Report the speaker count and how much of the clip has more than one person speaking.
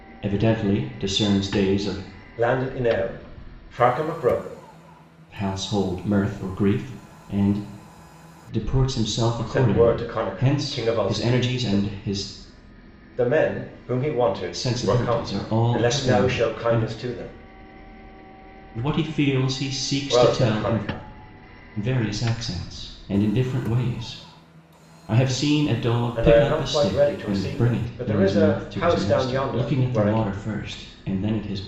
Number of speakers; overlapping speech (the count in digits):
2, about 29%